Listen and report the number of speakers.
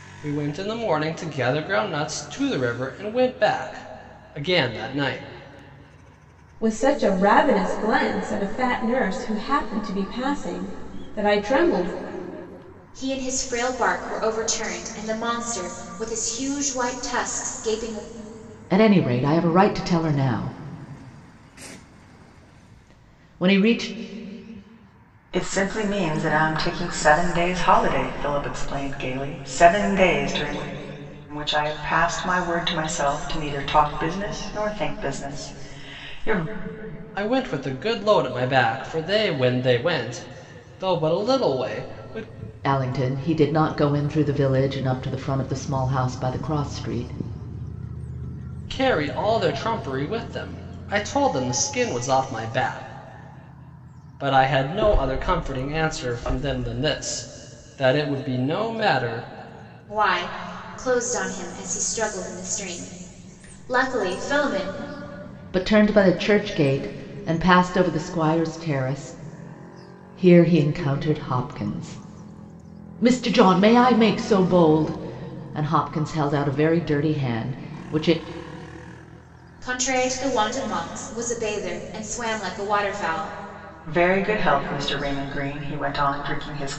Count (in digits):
5